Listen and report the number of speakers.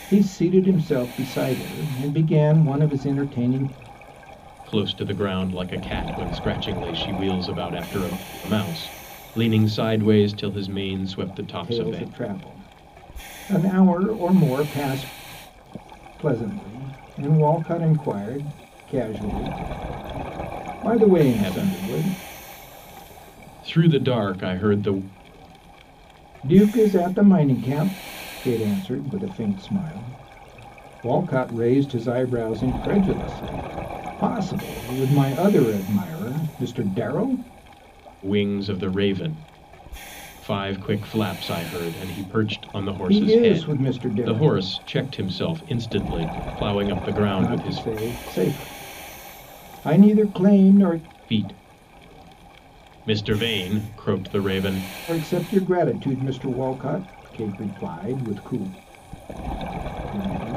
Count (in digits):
2